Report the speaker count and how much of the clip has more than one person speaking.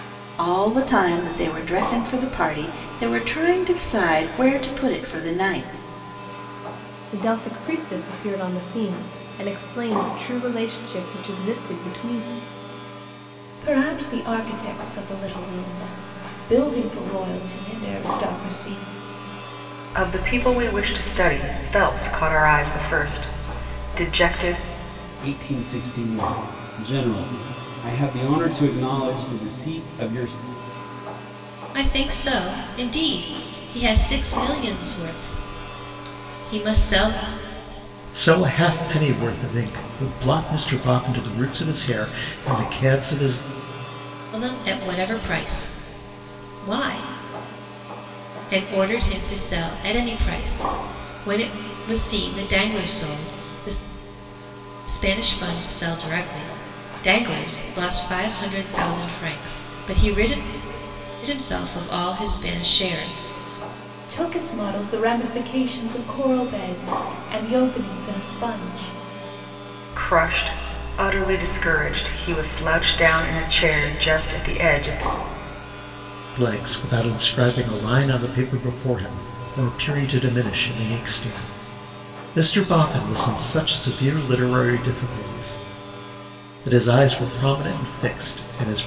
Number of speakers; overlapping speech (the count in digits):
7, no overlap